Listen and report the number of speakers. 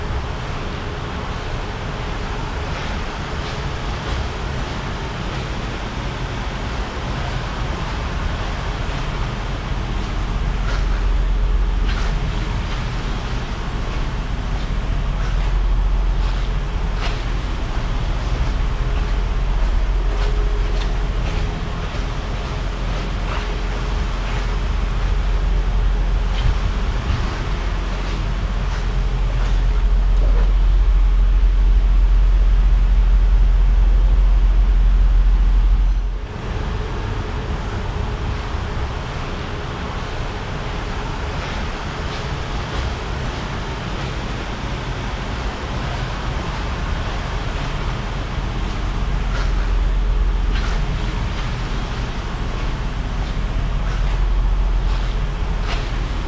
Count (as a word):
zero